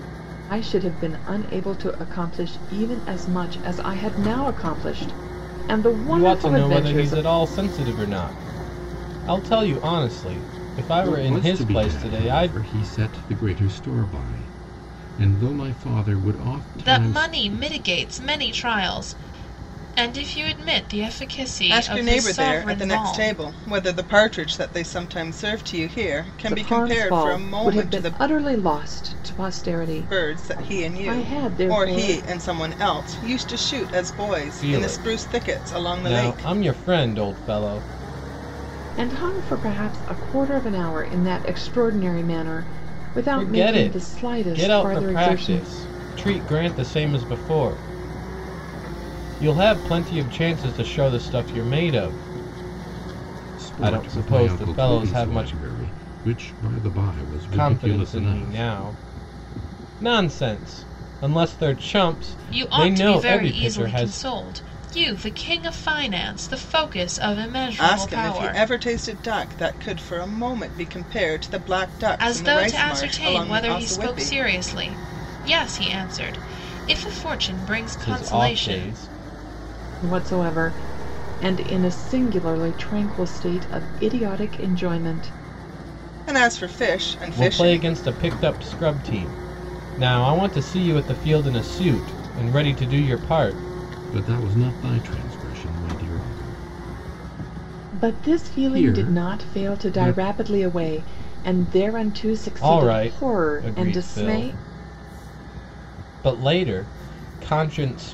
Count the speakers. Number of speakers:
five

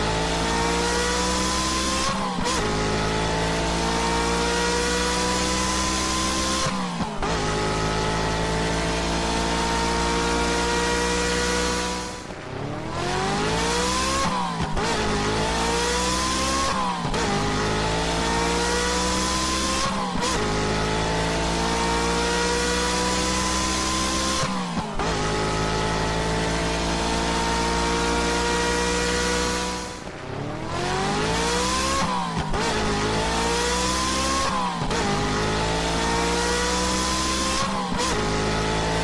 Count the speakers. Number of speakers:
zero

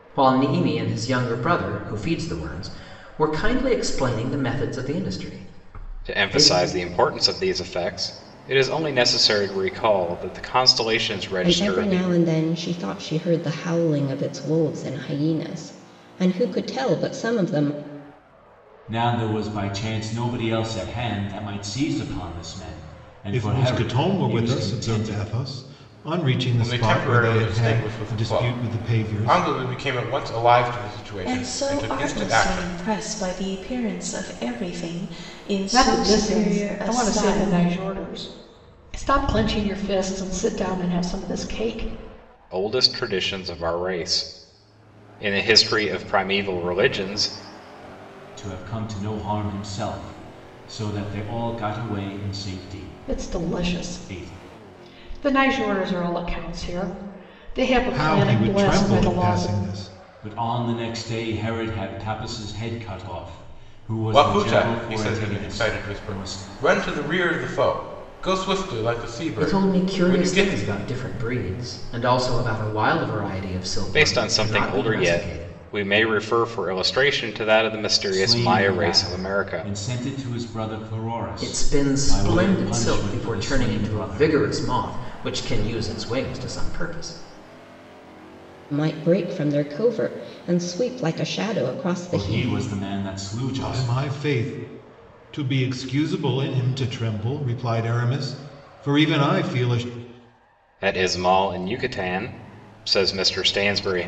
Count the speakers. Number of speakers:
eight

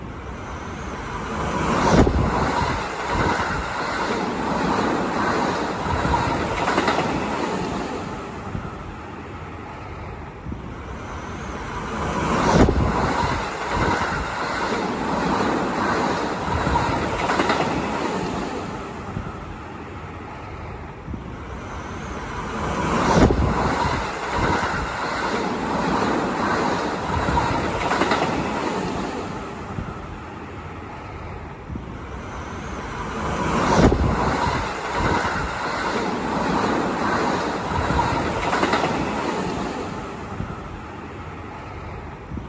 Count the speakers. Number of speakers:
zero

